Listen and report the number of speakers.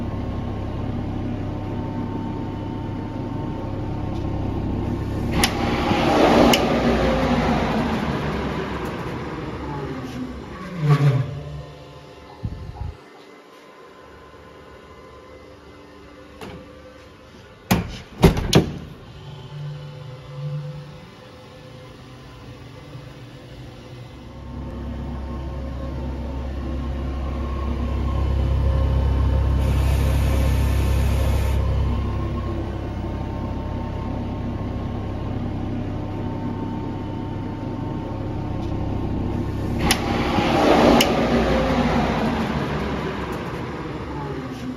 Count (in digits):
0